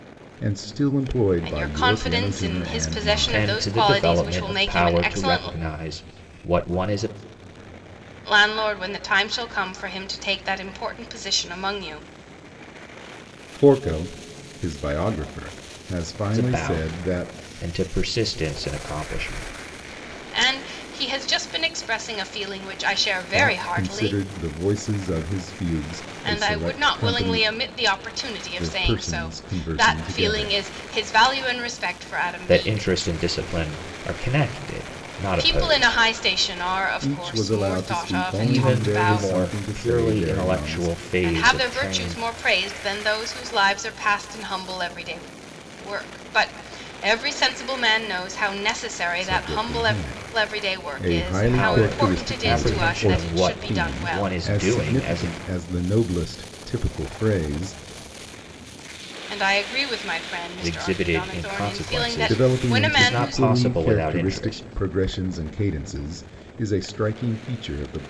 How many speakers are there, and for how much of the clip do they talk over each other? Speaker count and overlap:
three, about 37%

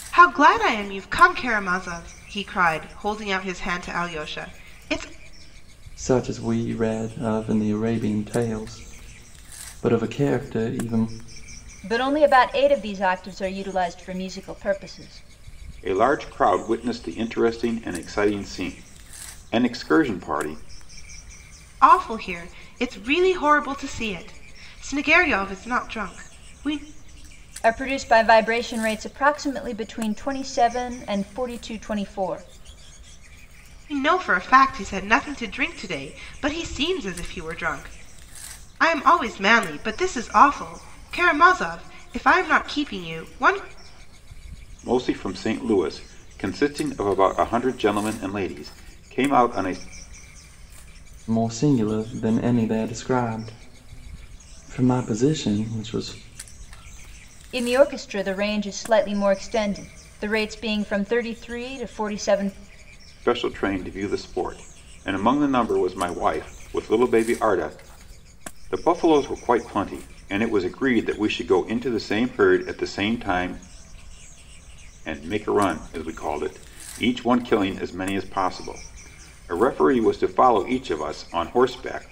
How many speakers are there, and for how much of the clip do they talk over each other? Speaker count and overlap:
four, no overlap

